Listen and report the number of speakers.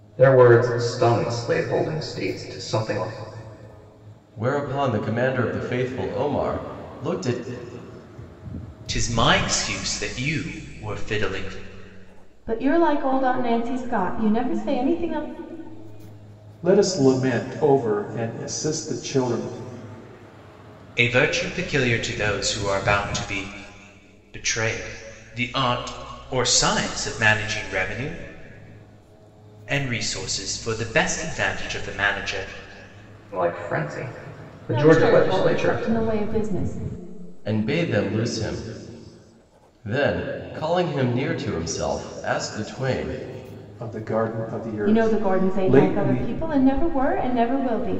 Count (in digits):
5